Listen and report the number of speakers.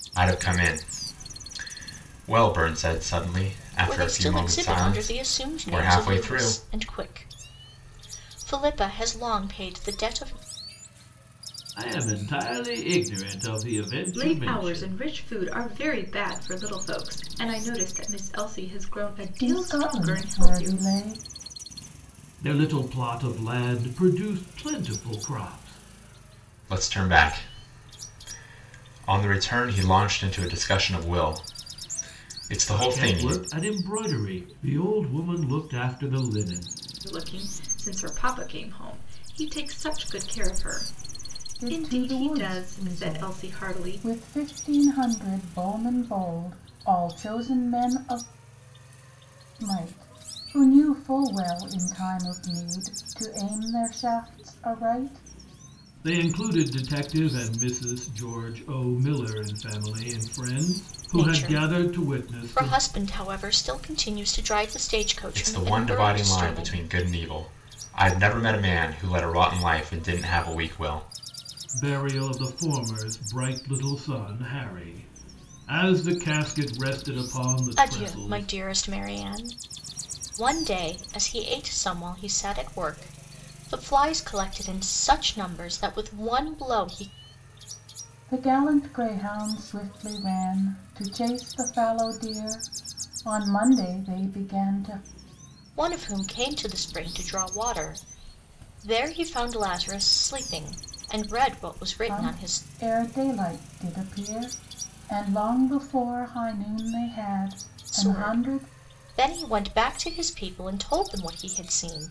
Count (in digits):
5